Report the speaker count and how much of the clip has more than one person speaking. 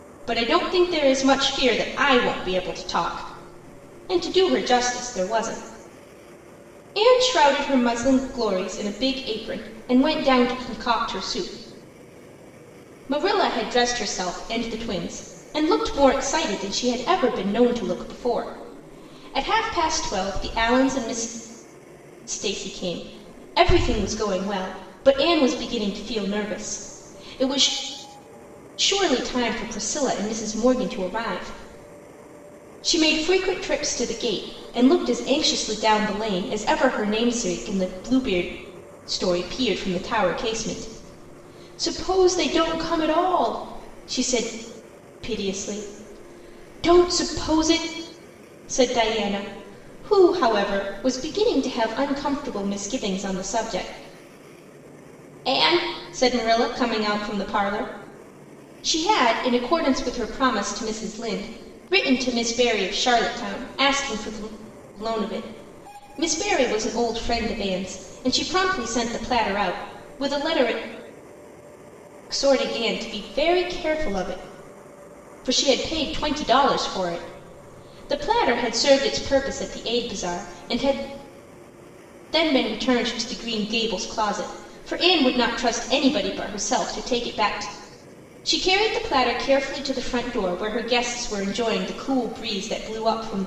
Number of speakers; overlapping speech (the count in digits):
1, no overlap